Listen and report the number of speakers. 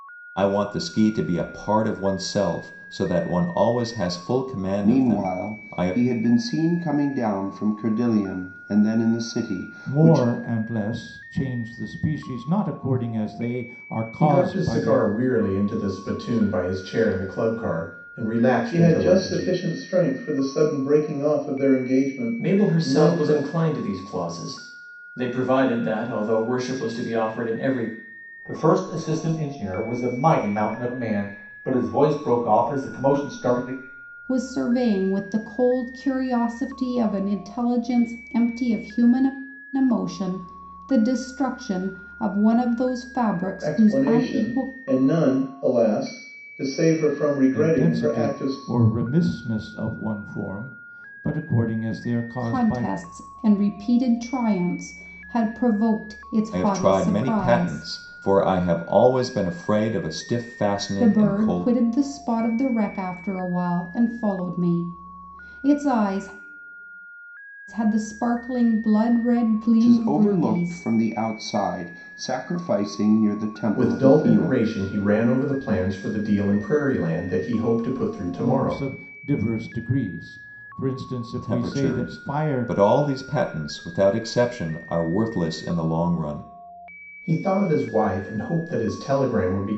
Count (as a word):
eight